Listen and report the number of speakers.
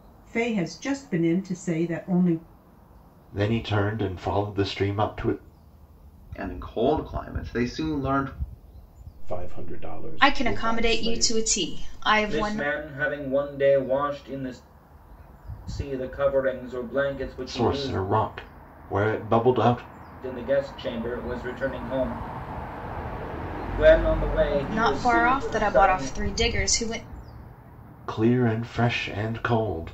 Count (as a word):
six